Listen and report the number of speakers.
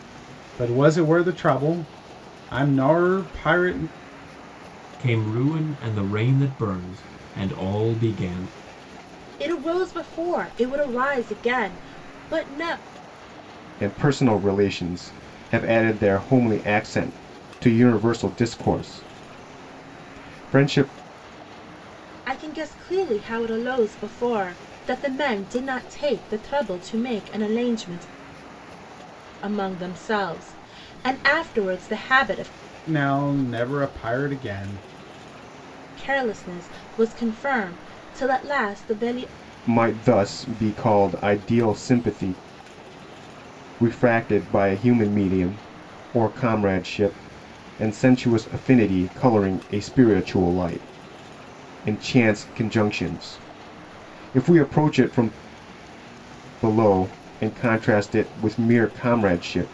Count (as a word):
four